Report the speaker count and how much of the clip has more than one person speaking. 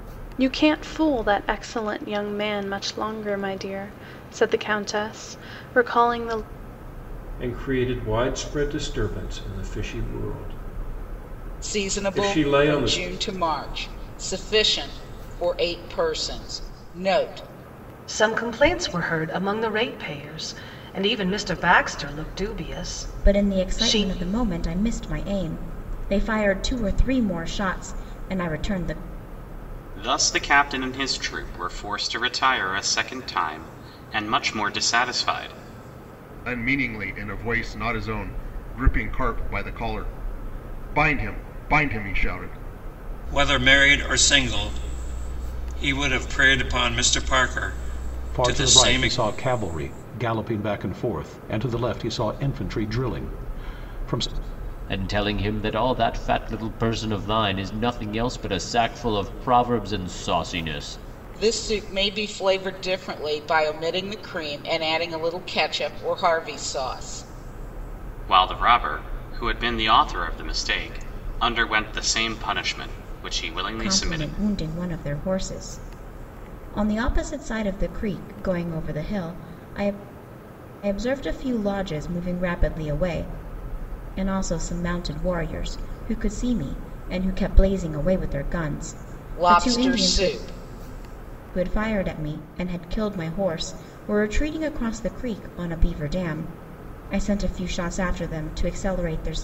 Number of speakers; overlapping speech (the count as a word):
ten, about 5%